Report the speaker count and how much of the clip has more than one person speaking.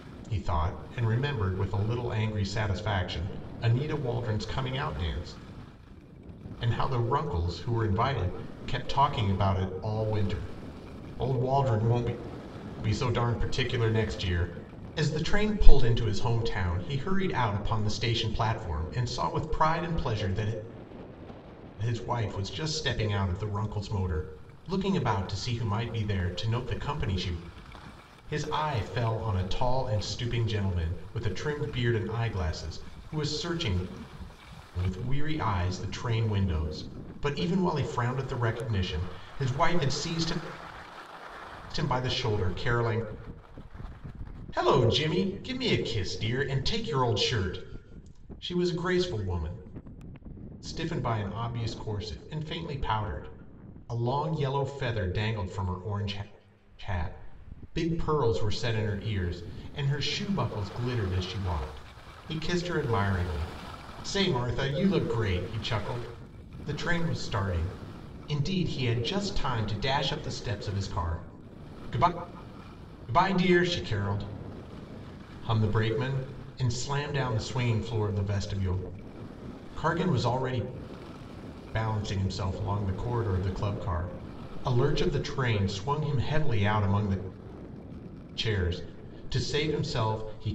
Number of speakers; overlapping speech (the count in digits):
1, no overlap